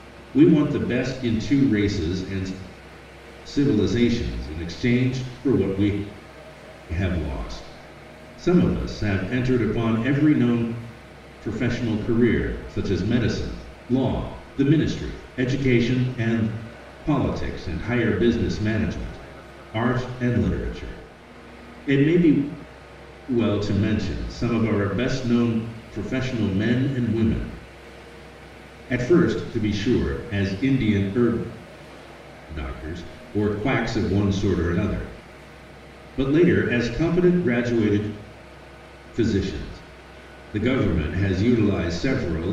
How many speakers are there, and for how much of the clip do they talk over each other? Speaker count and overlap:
one, no overlap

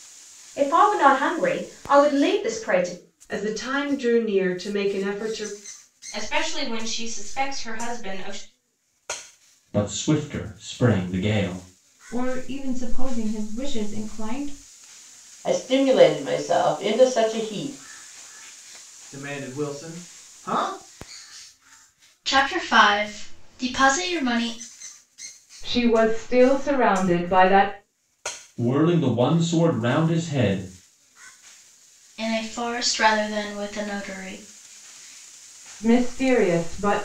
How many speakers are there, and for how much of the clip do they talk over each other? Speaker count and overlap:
nine, no overlap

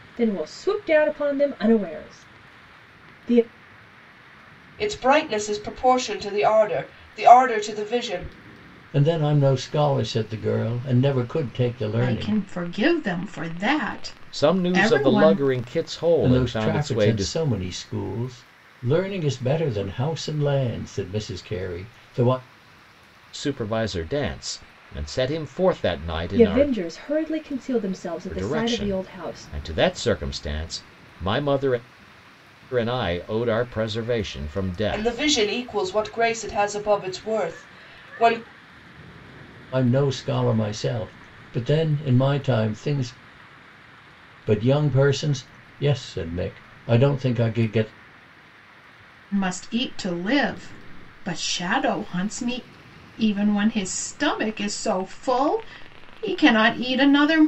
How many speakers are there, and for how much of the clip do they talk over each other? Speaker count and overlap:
five, about 8%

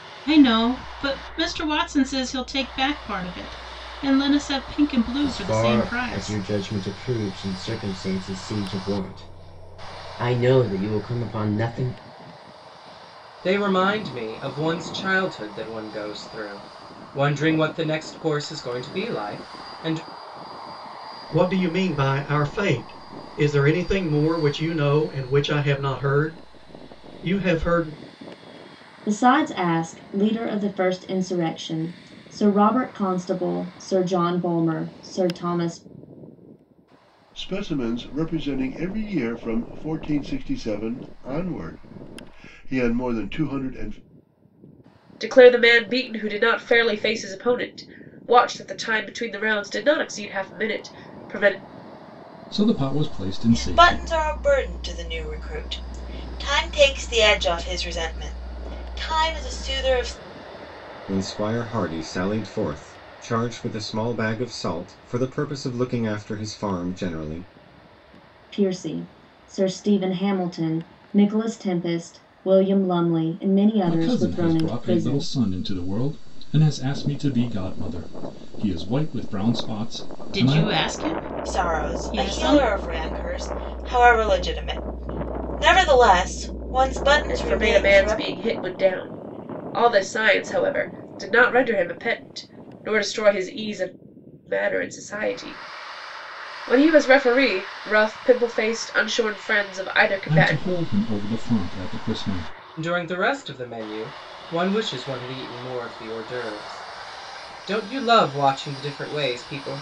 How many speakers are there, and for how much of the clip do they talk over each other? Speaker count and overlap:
ten, about 6%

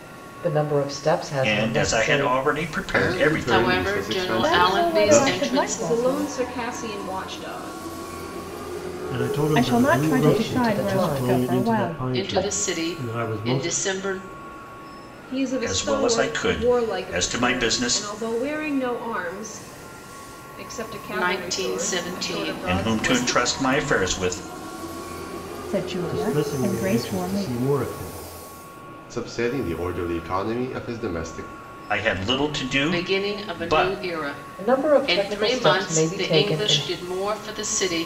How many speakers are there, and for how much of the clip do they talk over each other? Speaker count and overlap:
seven, about 47%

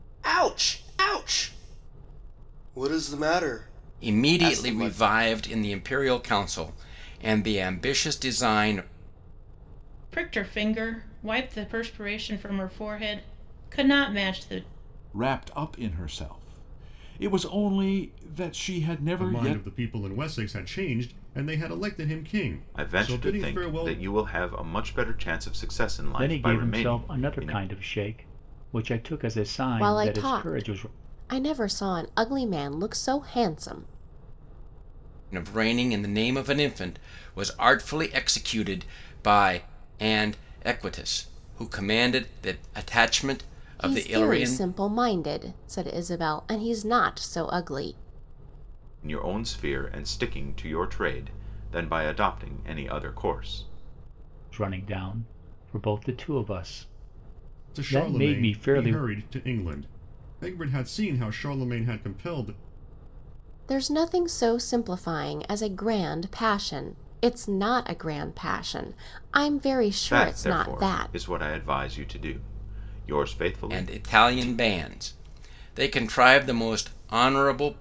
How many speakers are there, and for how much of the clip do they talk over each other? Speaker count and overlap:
eight, about 13%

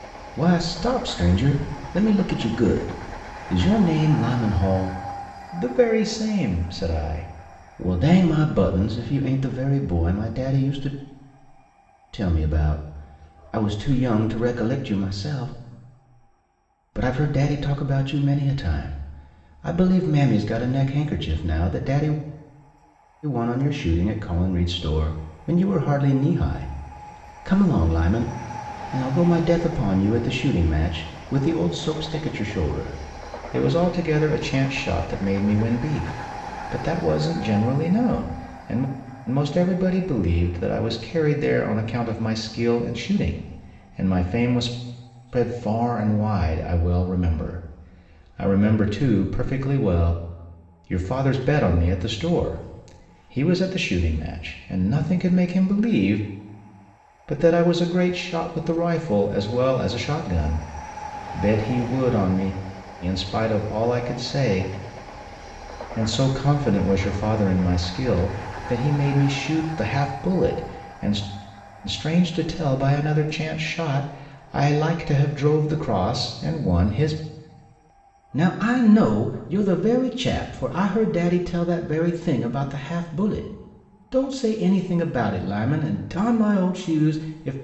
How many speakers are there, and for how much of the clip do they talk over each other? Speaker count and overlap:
one, no overlap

